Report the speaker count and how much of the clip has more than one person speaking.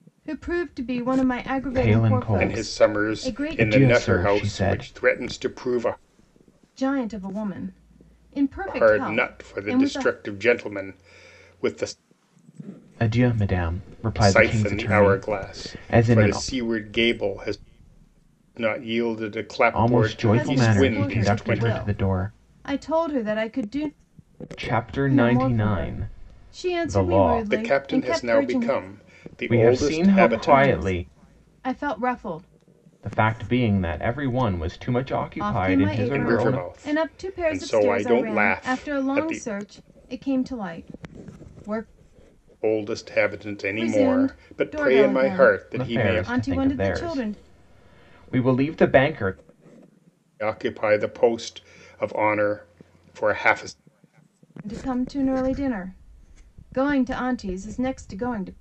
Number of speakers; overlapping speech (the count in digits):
3, about 38%